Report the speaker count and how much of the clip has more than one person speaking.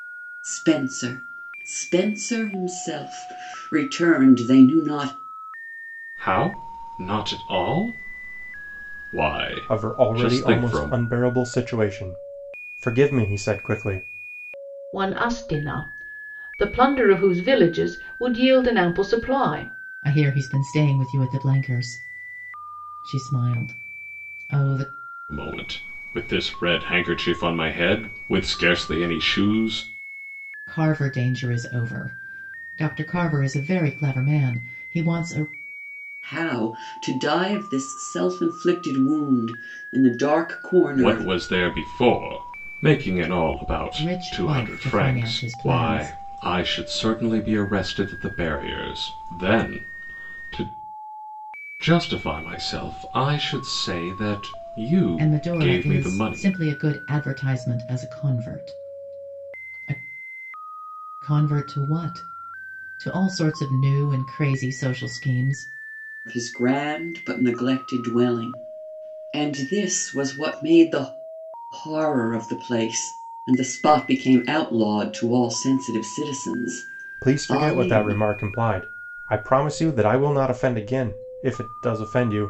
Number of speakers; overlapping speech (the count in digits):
5, about 7%